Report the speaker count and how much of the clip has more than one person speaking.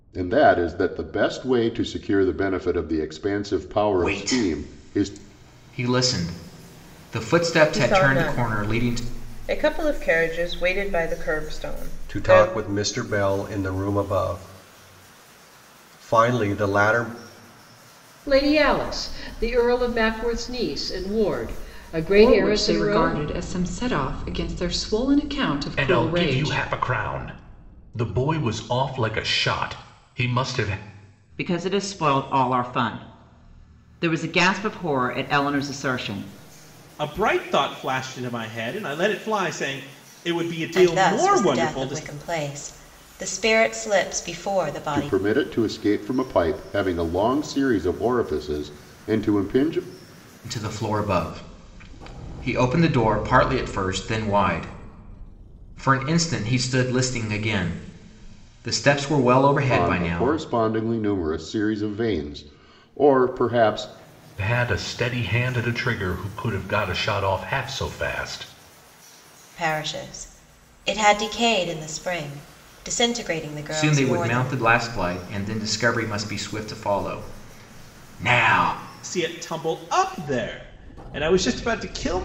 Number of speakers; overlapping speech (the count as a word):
ten, about 10%